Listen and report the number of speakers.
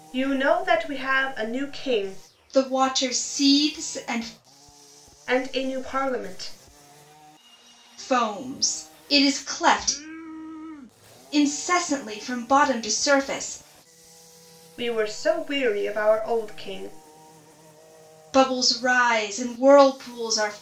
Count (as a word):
two